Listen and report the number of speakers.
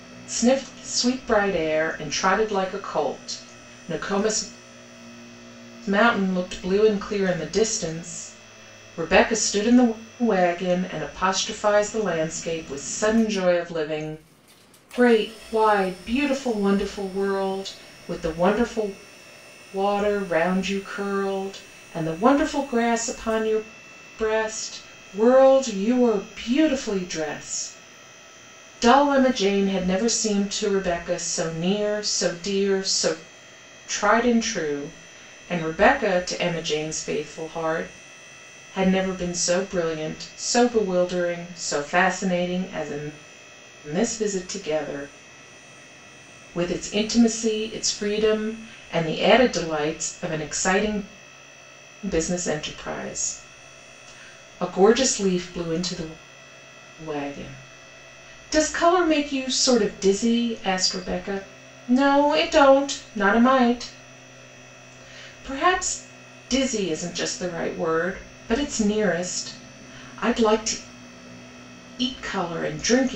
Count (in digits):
1